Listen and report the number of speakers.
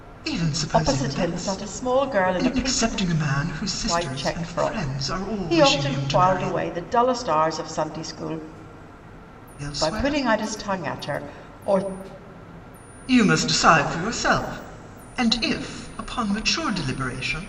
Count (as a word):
two